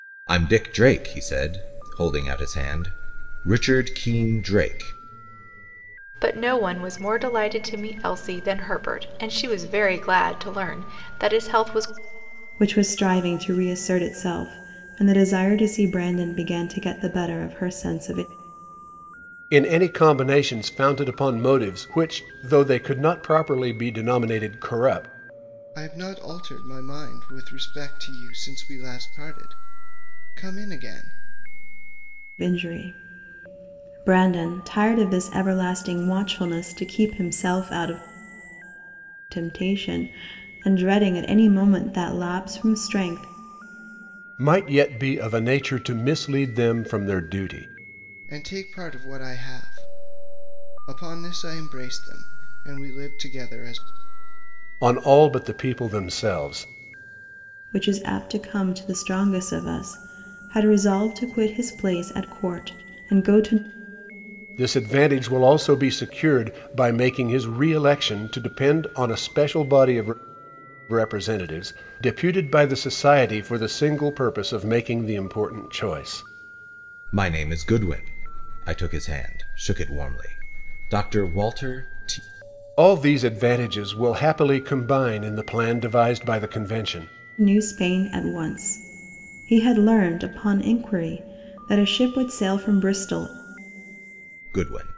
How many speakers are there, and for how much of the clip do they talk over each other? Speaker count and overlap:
5, no overlap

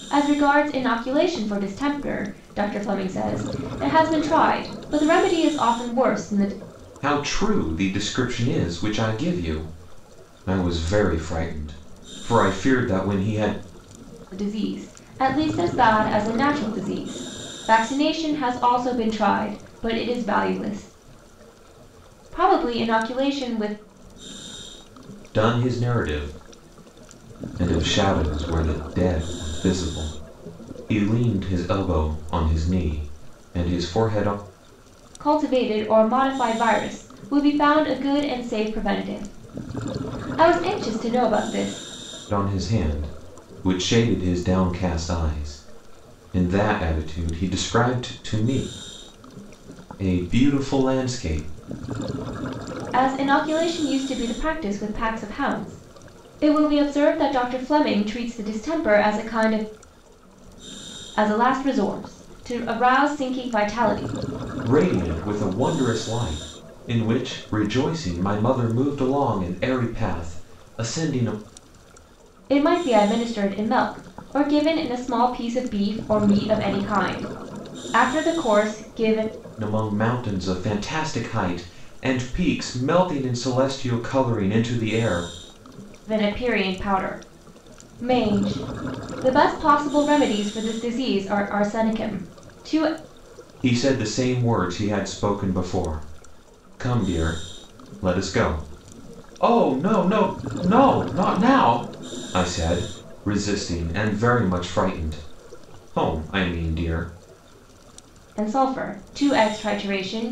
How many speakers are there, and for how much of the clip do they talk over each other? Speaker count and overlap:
2, no overlap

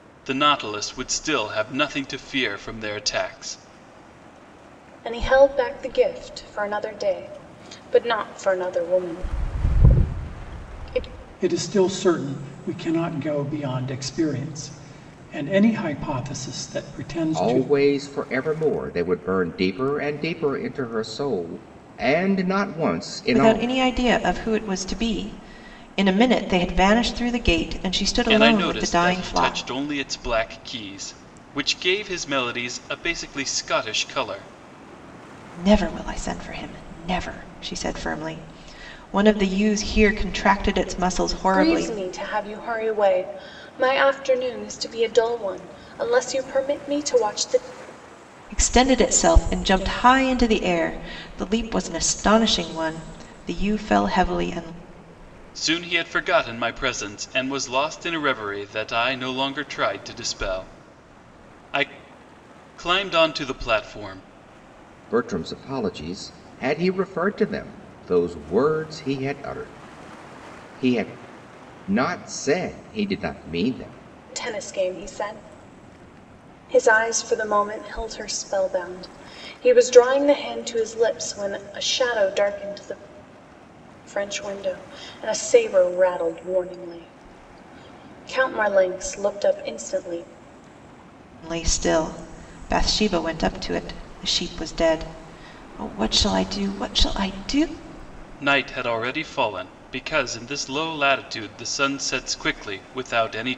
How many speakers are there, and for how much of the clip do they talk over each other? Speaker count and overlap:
5, about 3%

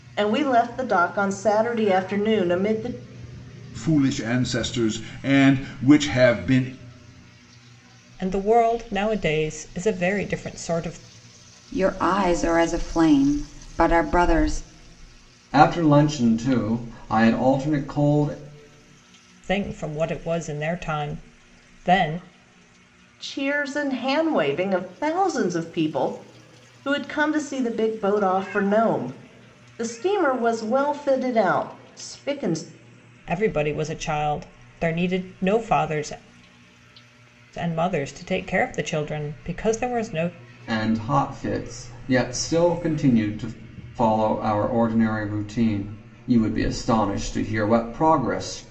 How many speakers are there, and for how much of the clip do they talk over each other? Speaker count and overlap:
5, no overlap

